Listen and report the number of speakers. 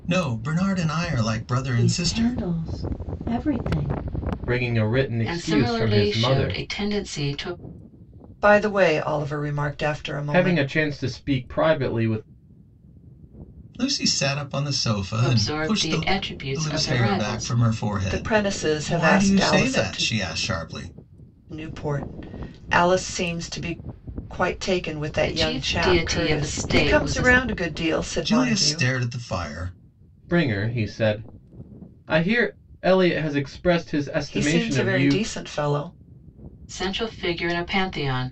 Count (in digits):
5